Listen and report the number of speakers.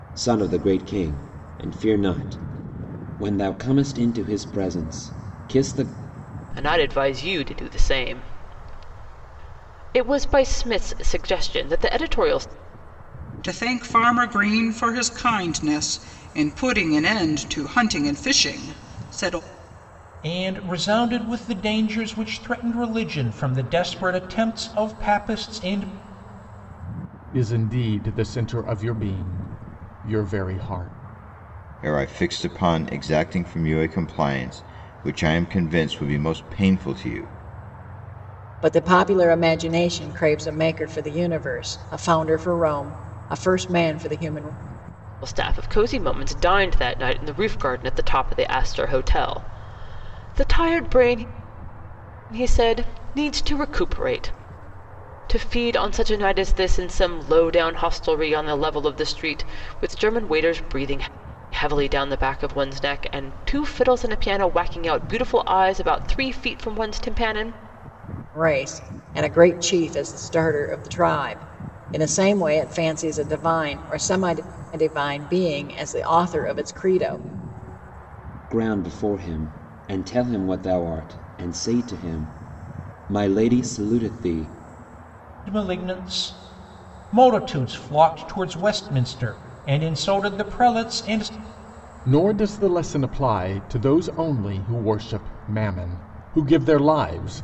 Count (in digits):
7